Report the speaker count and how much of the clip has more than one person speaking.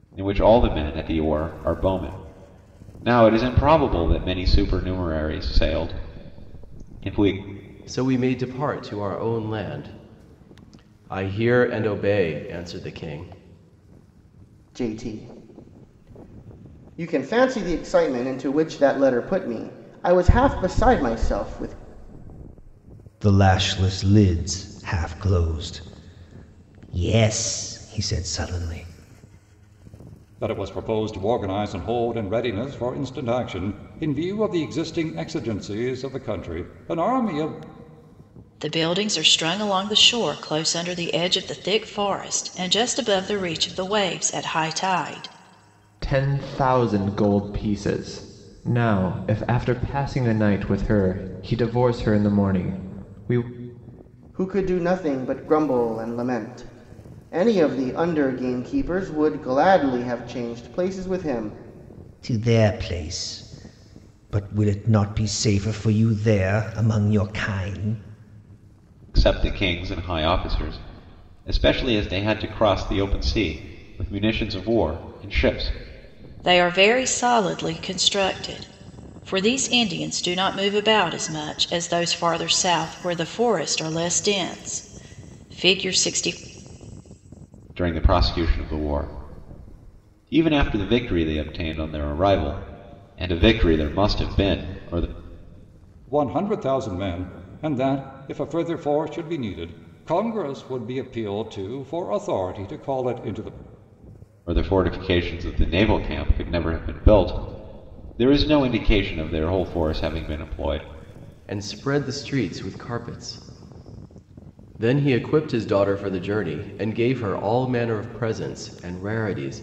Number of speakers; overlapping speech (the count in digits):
7, no overlap